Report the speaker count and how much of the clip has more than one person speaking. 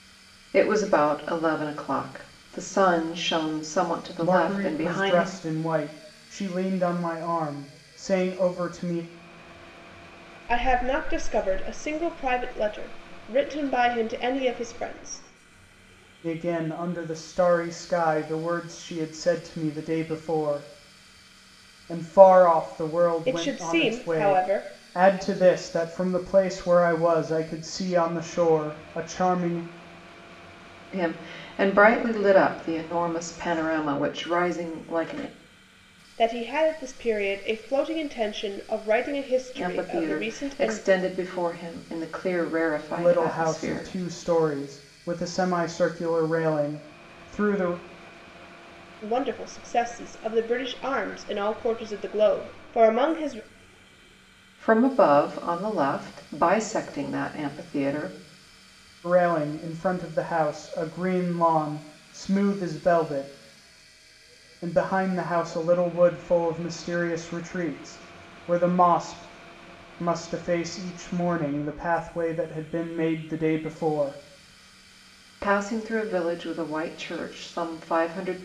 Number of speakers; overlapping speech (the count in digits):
3, about 6%